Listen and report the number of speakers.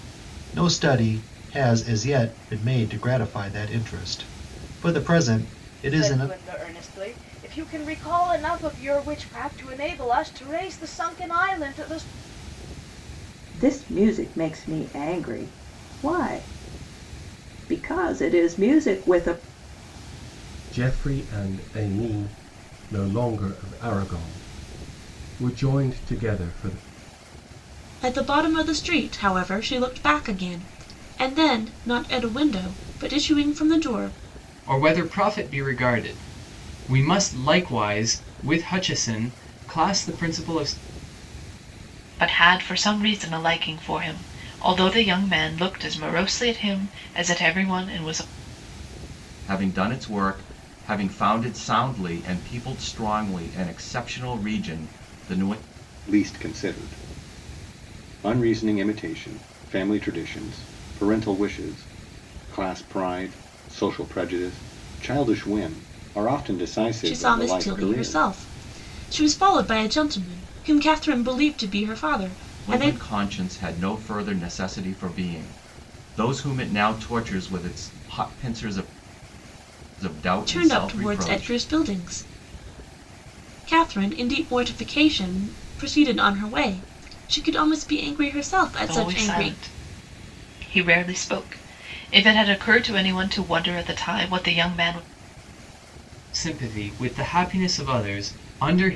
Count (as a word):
nine